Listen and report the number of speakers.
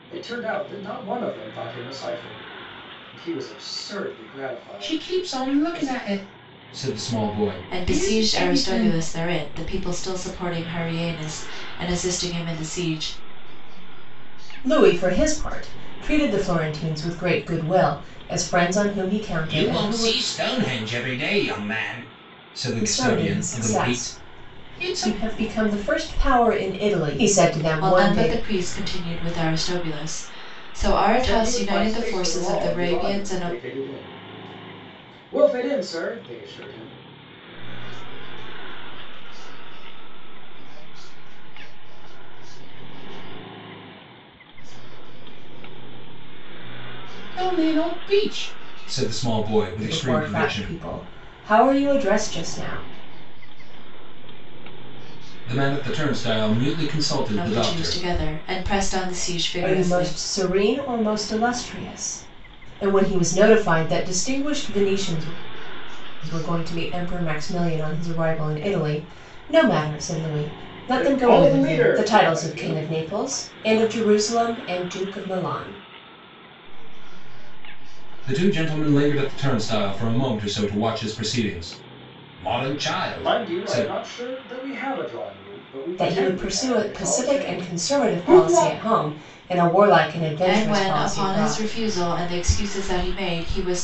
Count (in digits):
5